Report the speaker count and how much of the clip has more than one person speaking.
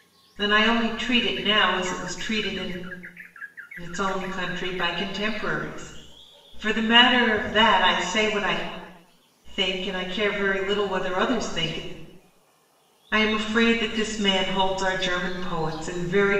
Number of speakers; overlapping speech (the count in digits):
1, no overlap